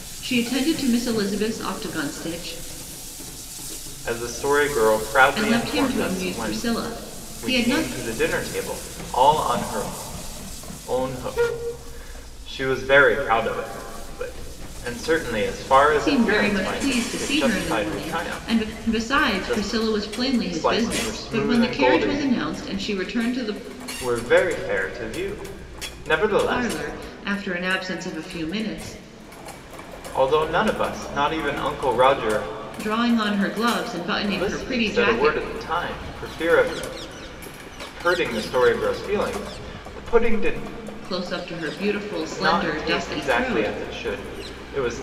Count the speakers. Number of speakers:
two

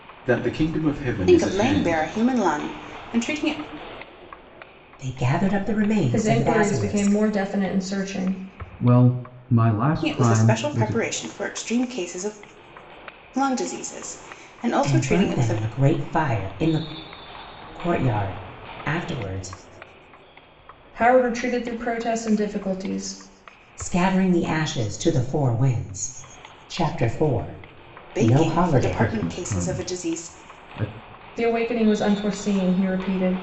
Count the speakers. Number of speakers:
five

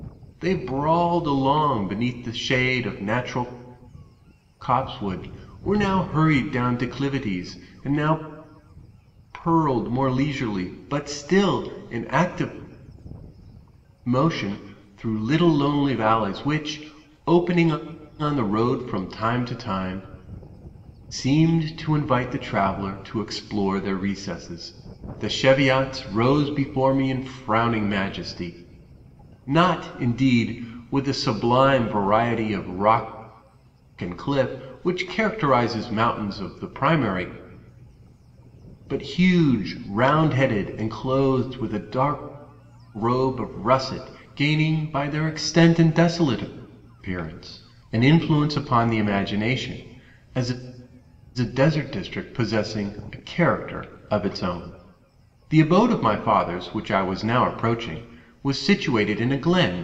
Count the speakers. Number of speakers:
one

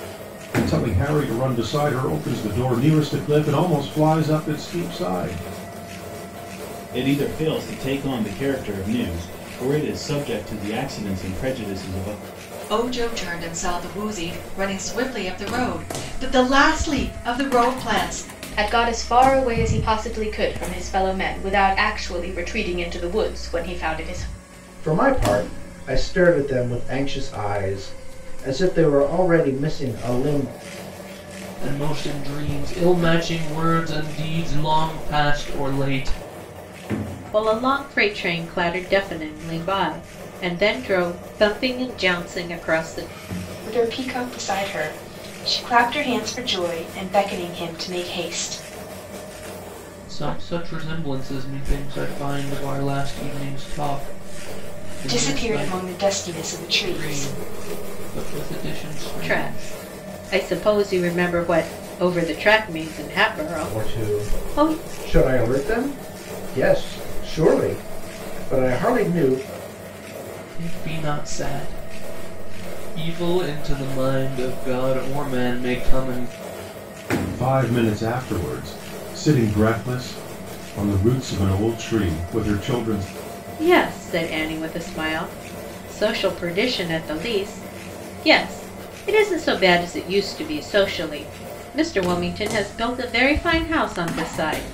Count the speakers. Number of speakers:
eight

